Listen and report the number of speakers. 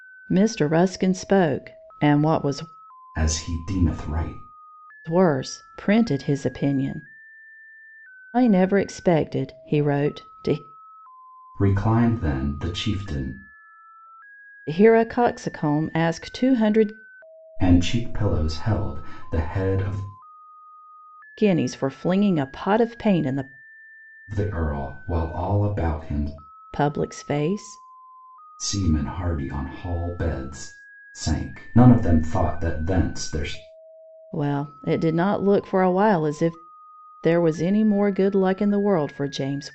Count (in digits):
2